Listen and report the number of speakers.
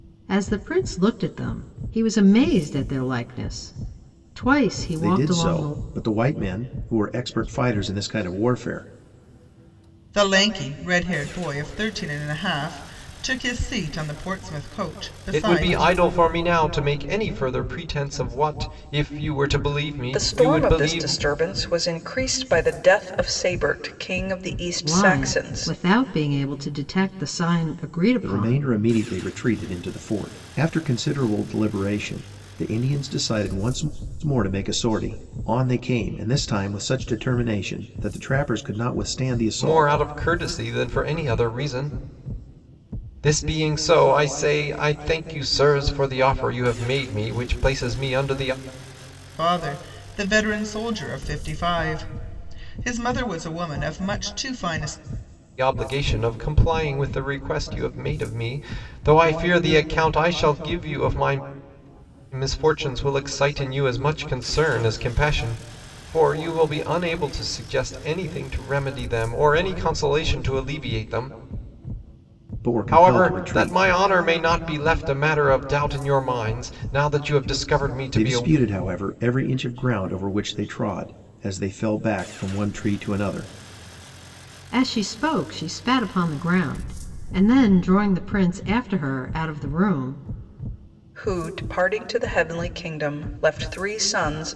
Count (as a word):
five